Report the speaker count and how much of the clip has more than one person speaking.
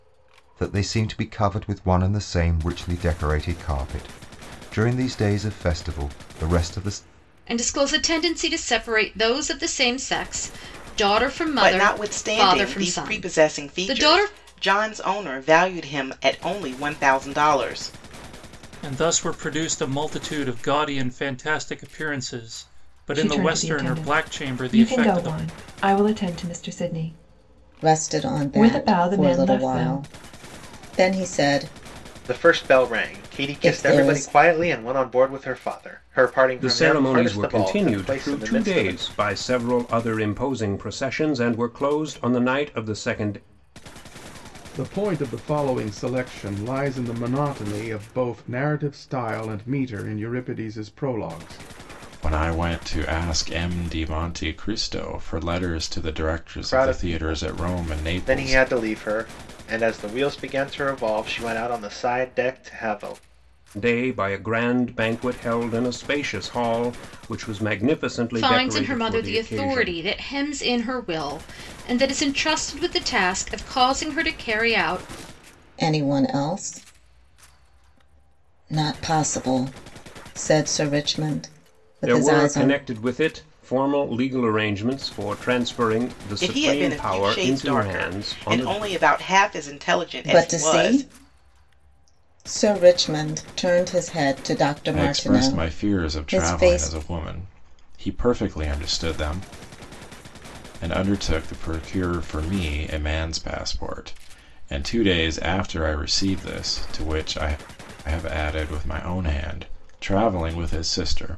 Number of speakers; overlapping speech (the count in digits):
10, about 19%